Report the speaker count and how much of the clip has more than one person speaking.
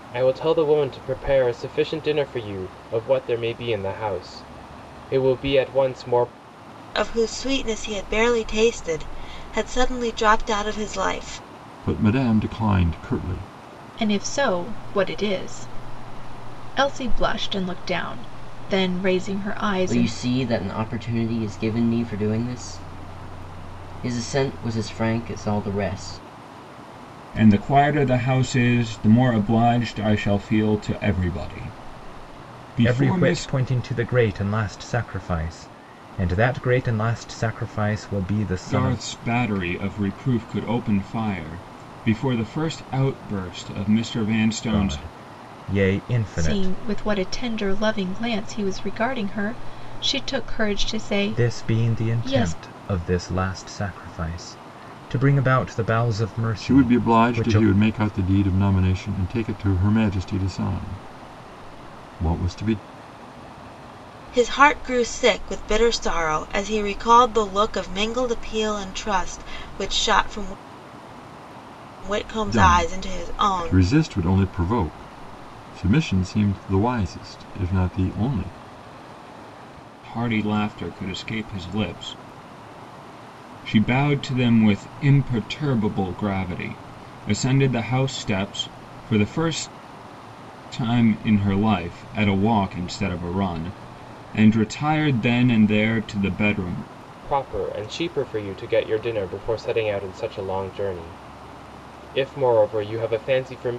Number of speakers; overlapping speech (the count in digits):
7, about 6%